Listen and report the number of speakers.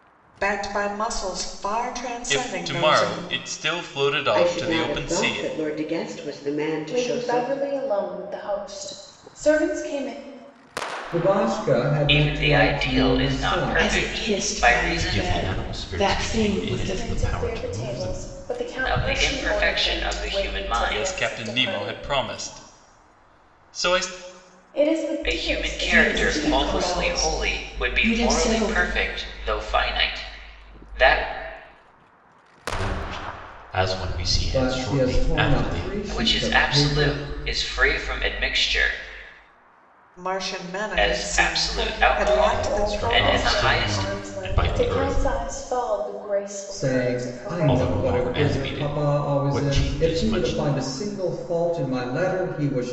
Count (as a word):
eight